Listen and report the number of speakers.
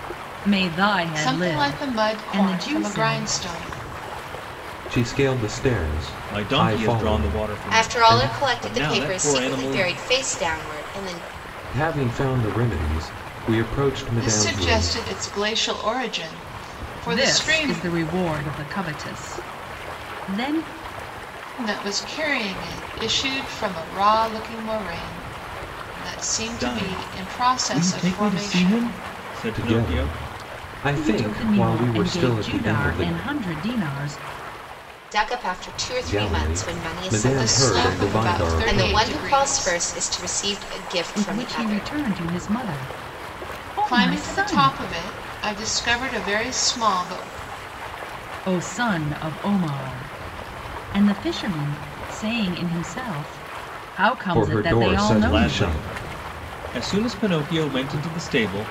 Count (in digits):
5